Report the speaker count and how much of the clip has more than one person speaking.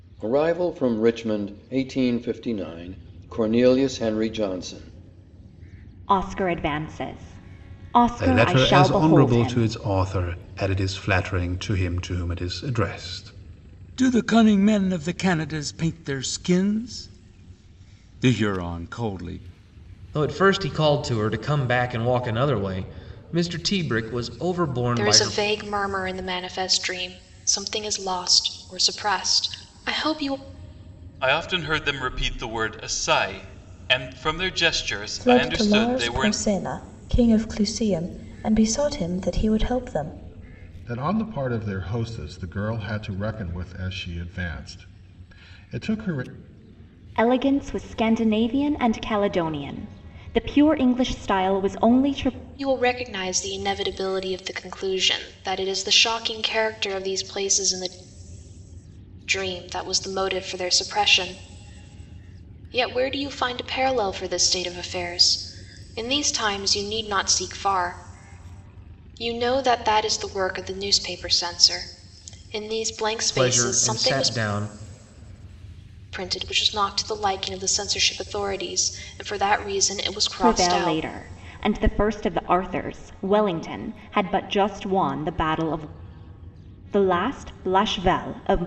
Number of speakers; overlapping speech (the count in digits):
9, about 6%